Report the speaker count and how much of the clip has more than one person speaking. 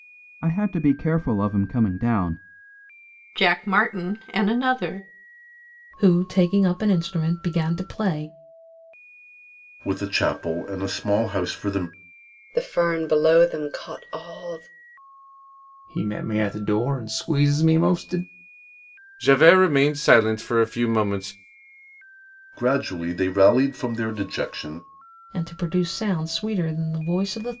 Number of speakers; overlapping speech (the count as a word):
seven, no overlap